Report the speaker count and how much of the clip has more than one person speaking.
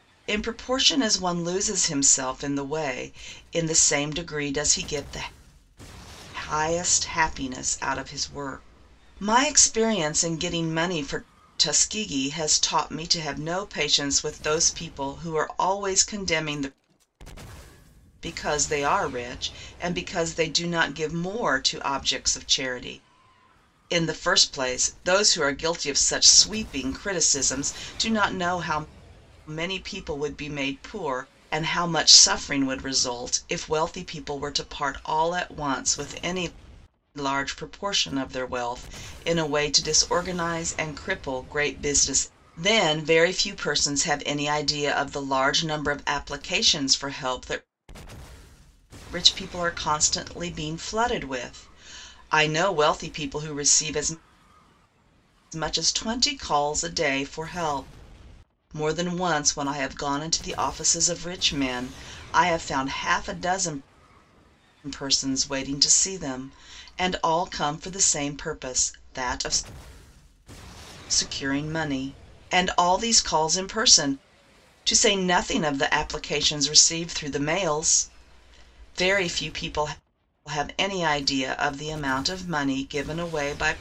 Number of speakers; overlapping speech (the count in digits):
1, no overlap